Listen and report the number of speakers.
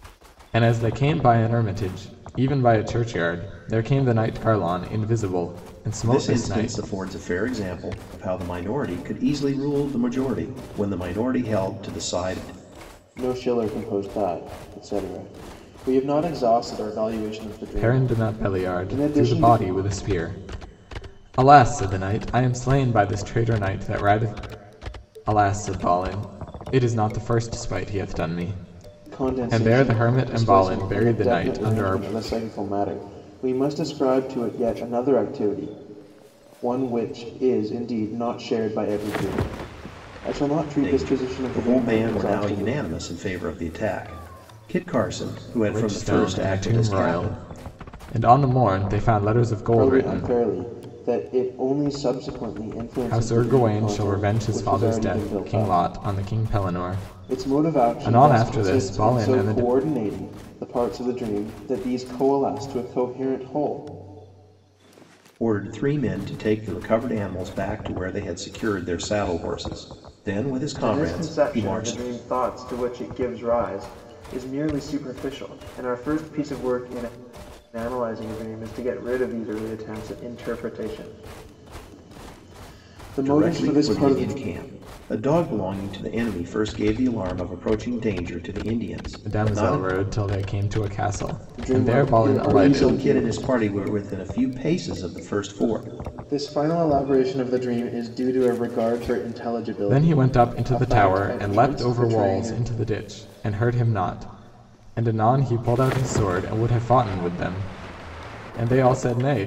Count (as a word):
three